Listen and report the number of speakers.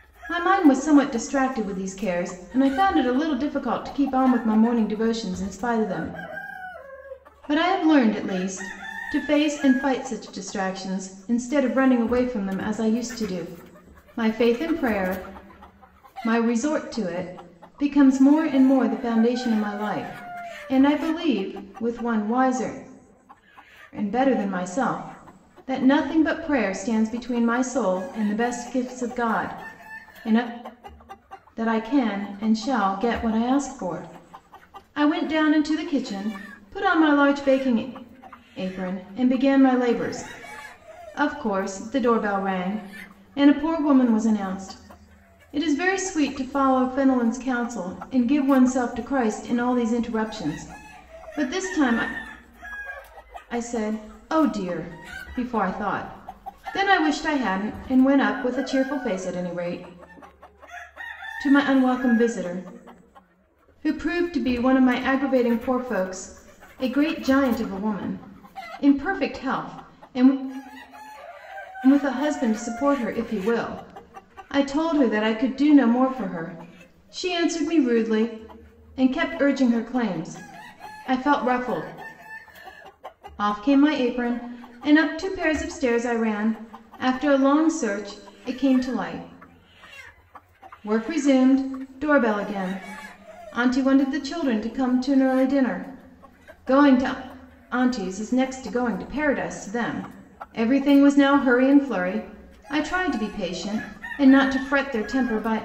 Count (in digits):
1